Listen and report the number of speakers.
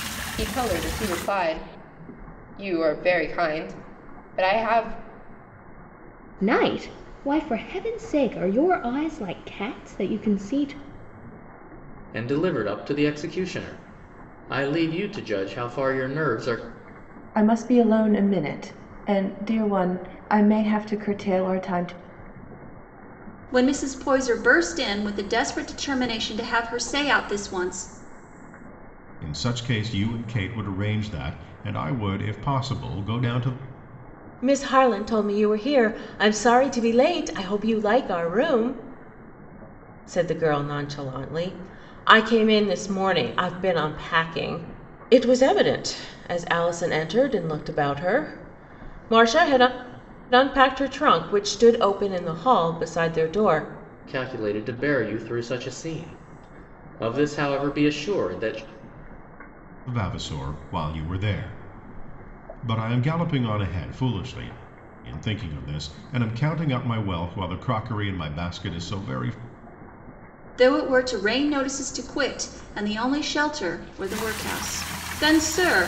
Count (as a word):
seven